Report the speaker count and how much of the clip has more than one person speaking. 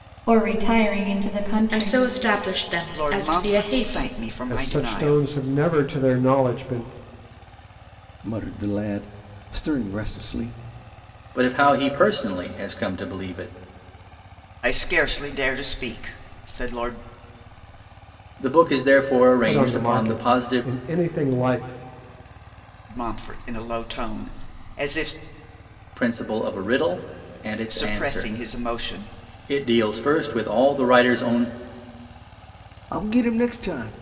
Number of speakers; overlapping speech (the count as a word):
six, about 13%